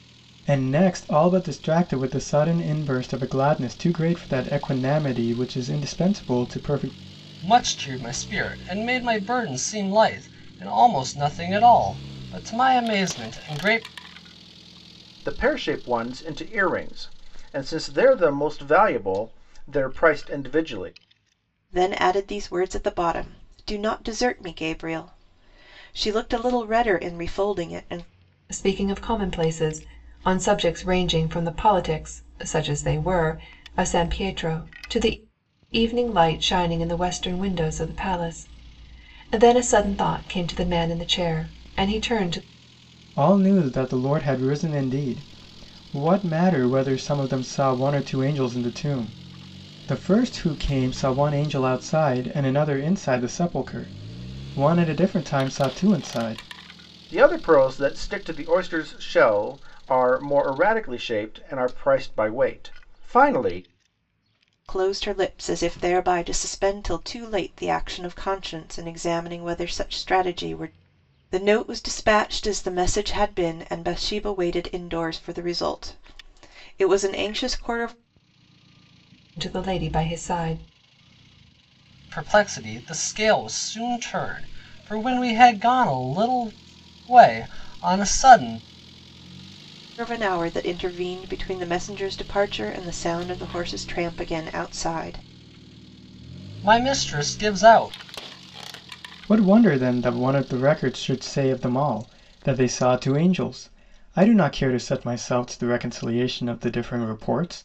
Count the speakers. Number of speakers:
five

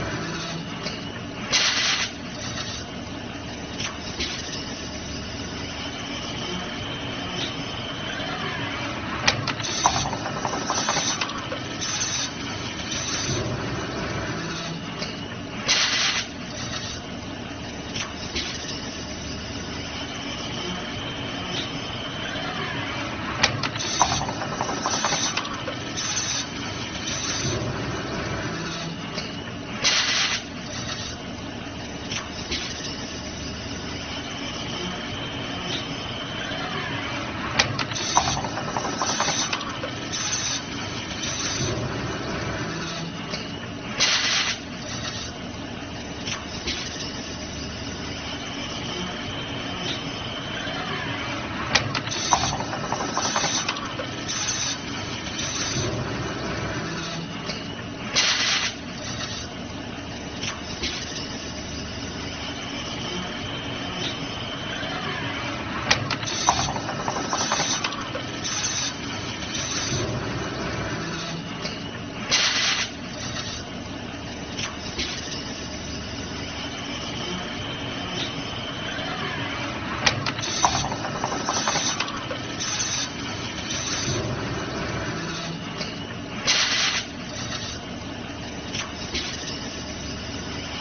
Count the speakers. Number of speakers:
zero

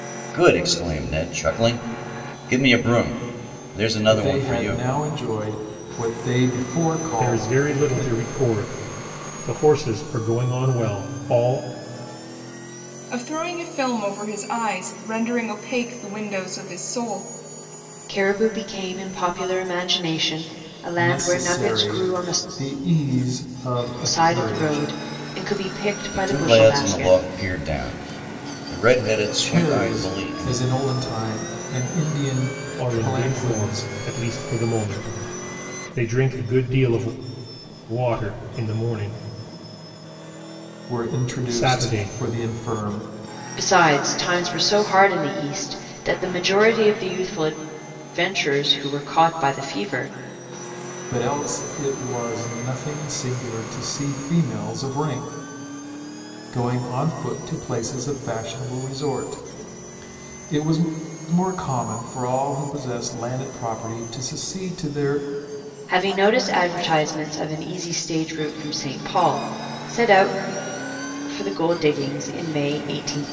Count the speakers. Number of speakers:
five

